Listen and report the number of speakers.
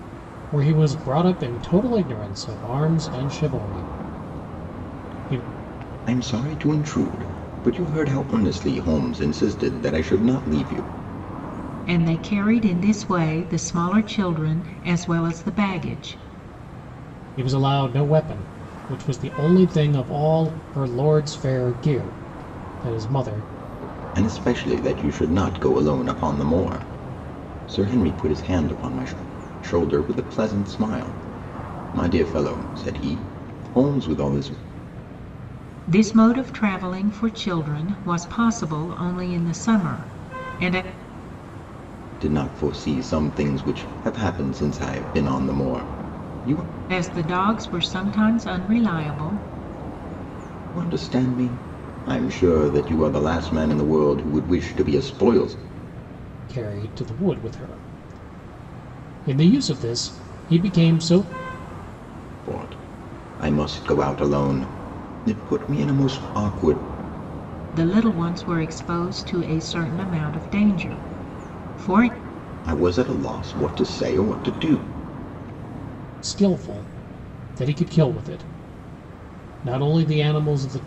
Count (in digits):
3